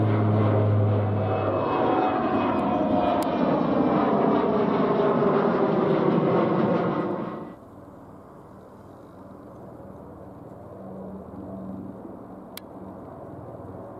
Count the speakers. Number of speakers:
zero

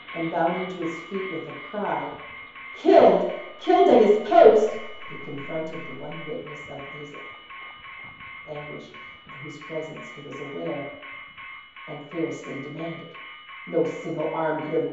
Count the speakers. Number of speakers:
one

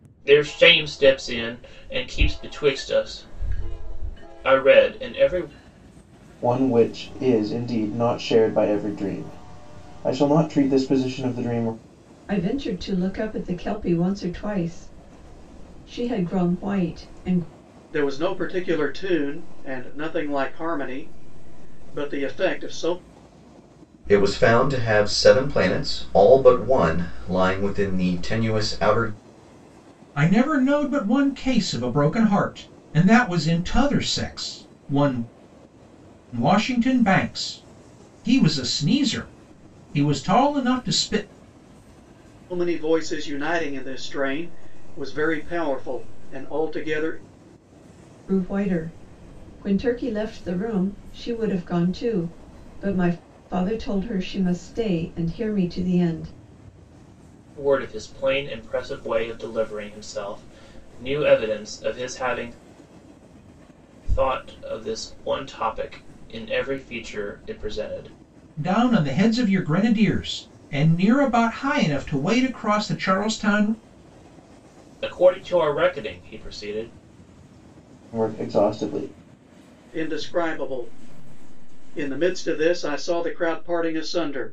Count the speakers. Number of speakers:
six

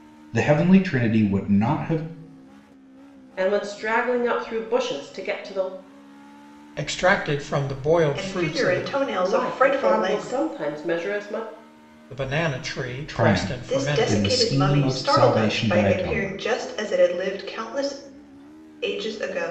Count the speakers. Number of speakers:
four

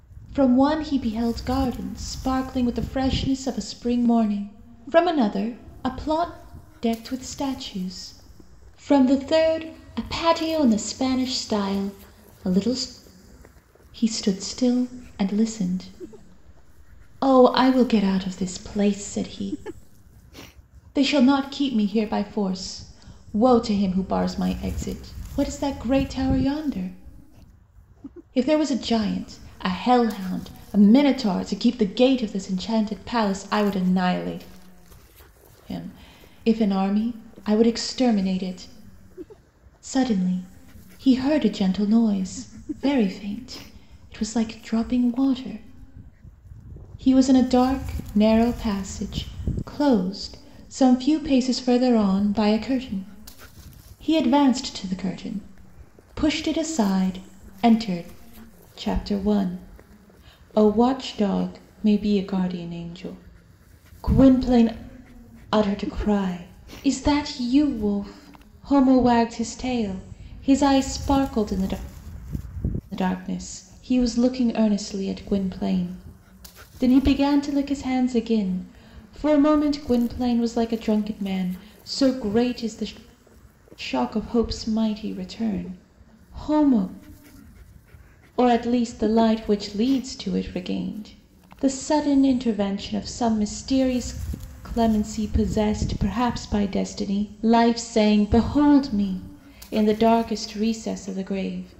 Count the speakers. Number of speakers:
one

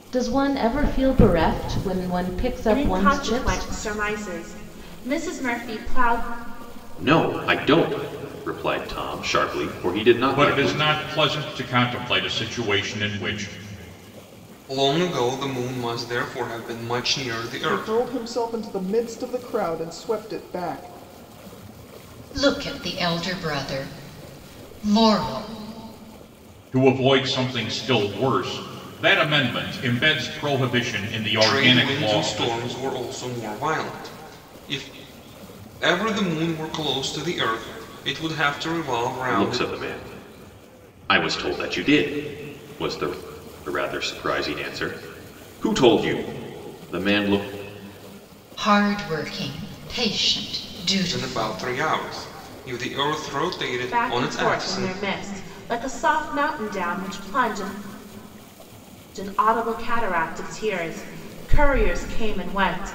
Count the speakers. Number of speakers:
seven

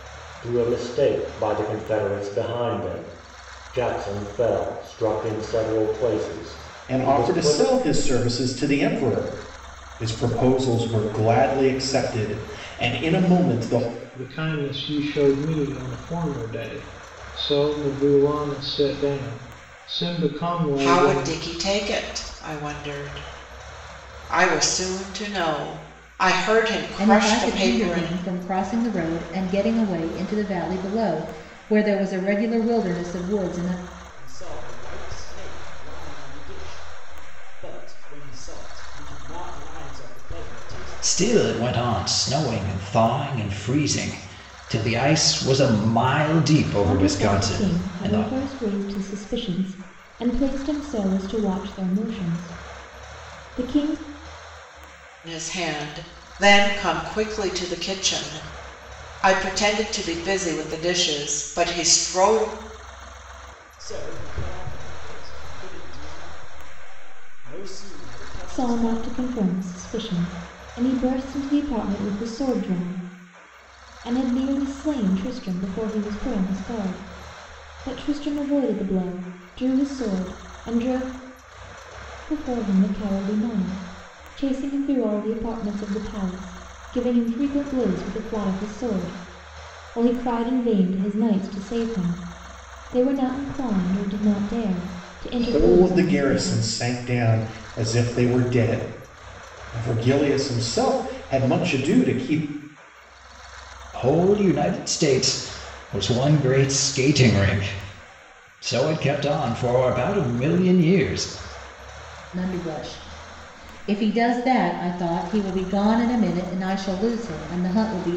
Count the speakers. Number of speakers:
eight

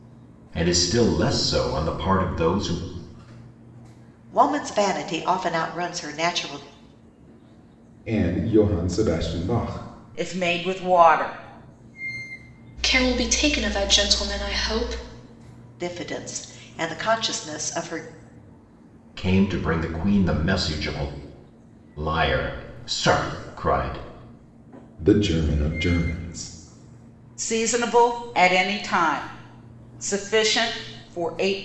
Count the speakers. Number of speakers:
five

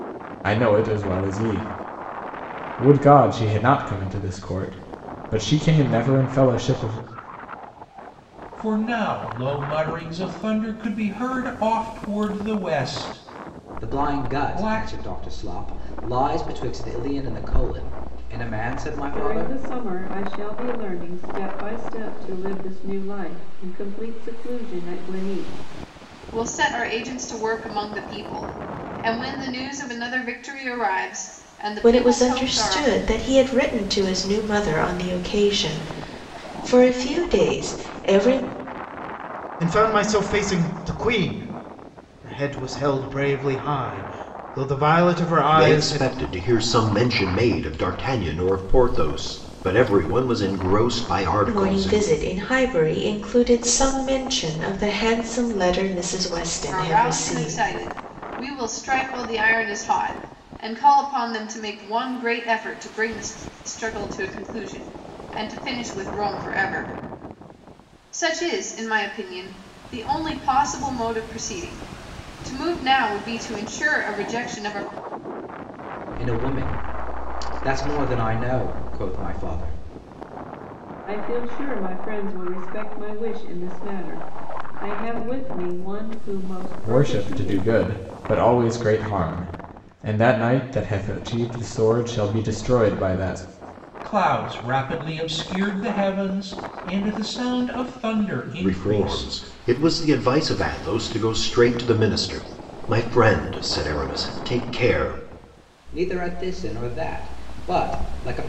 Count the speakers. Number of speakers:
eight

